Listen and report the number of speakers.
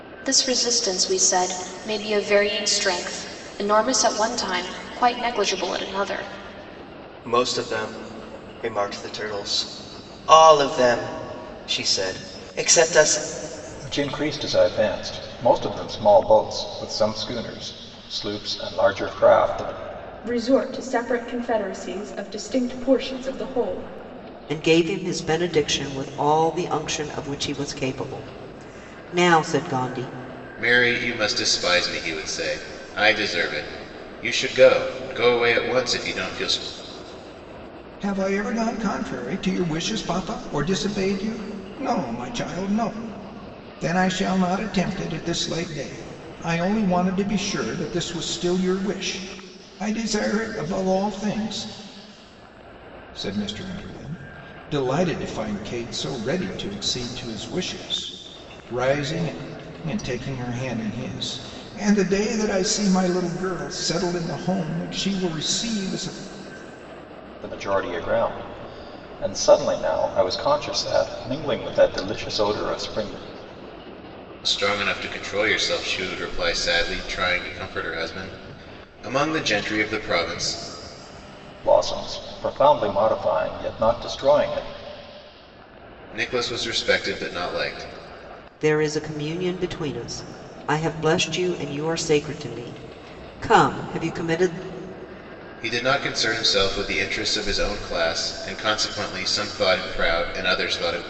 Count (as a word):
seven